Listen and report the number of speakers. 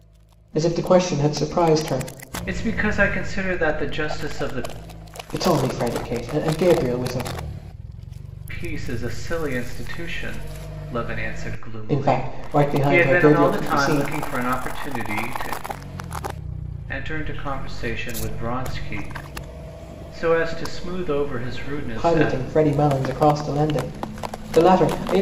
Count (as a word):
two